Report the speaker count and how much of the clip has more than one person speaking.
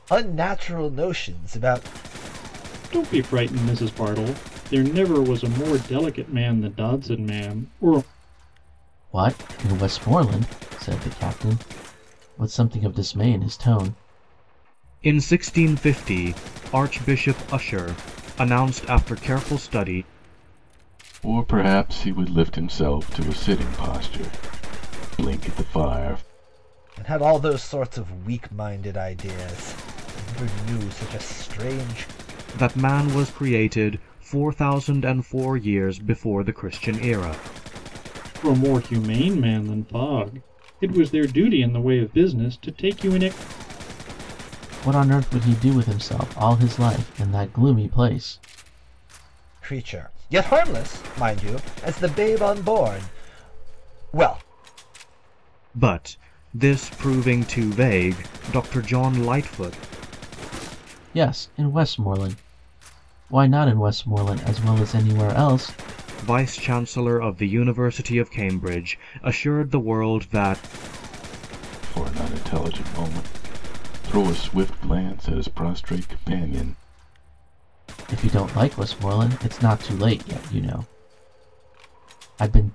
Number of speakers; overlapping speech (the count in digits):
5, no overlap